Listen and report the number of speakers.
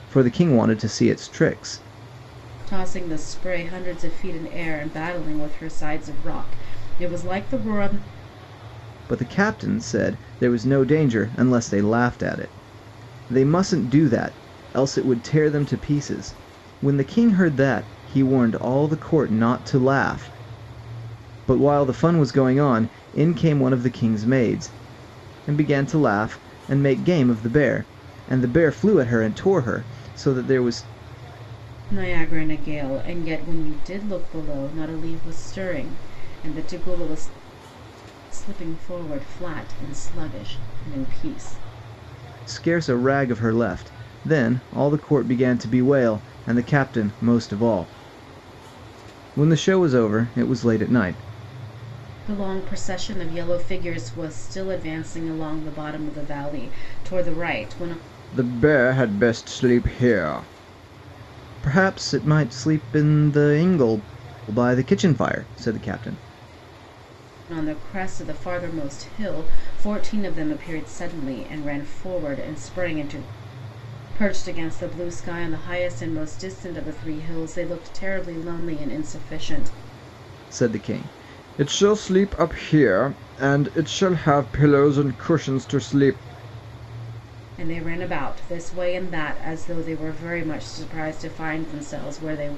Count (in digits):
2